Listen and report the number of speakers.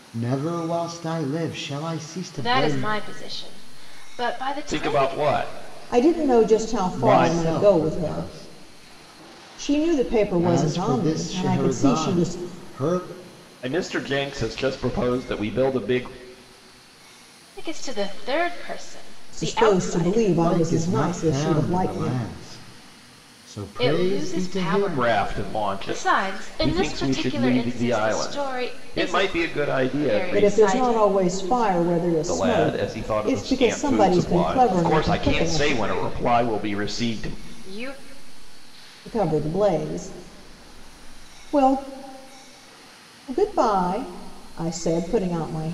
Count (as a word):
four